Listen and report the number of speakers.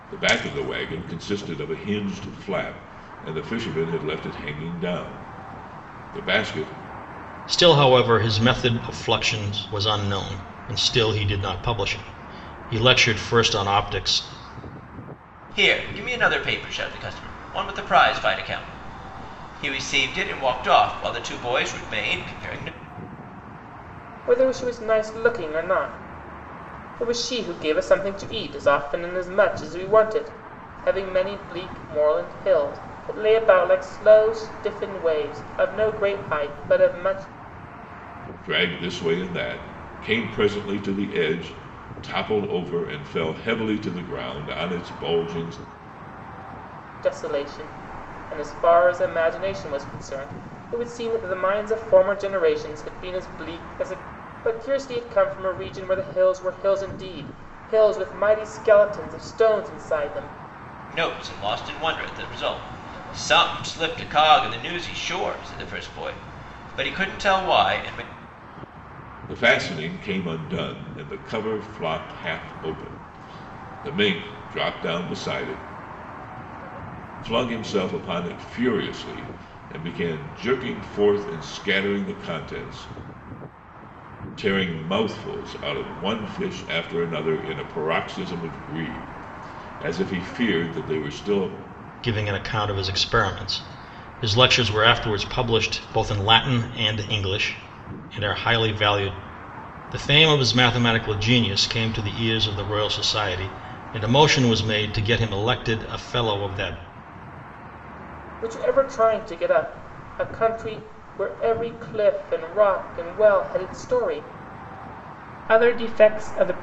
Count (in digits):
4